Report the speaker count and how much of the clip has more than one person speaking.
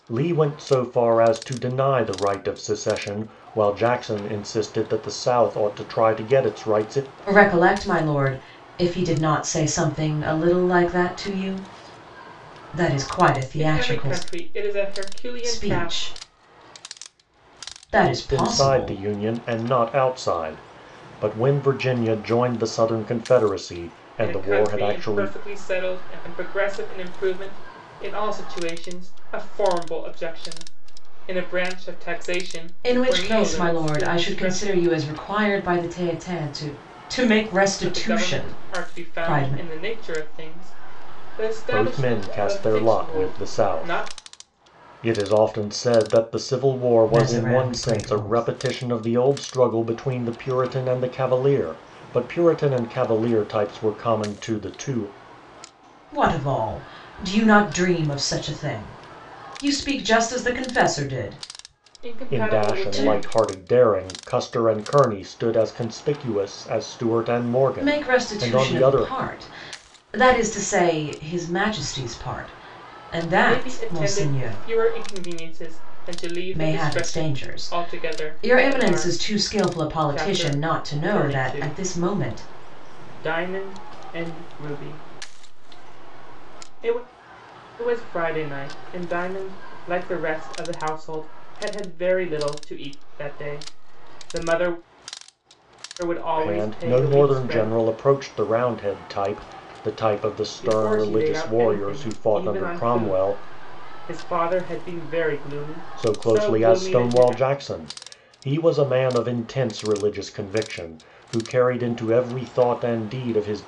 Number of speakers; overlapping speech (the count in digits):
3, about 23%